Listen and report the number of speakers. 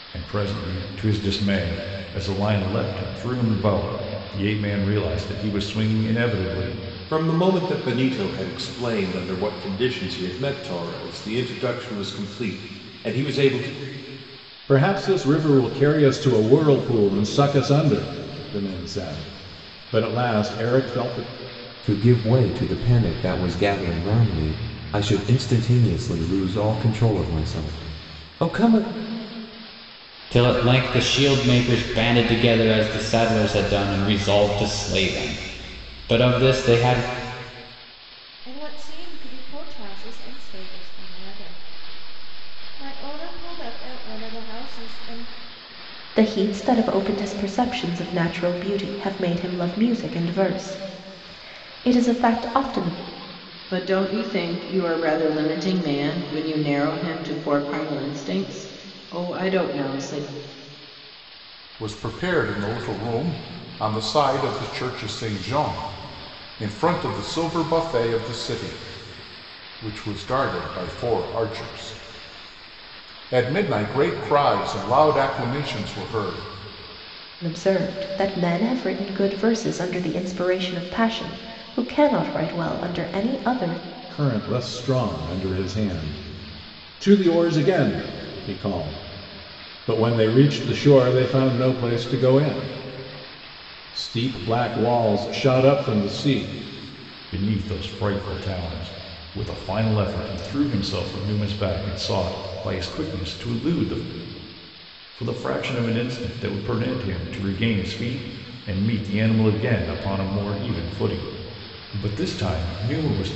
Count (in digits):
9